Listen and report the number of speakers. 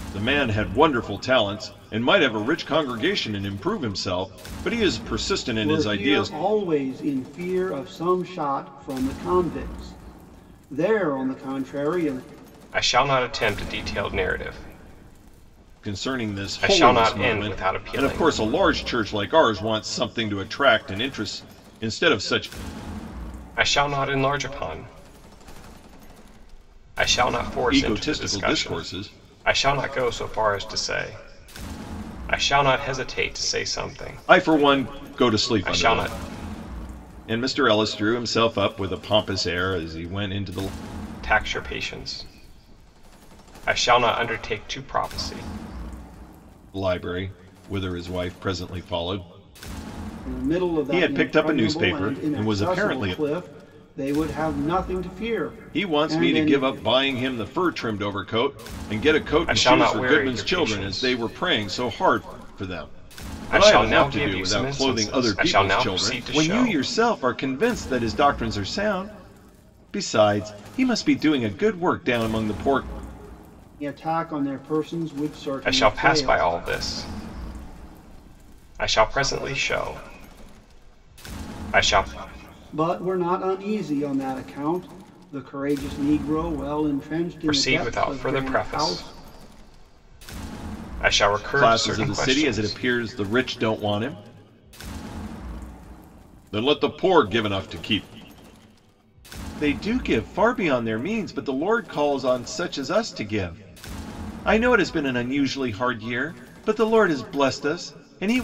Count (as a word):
three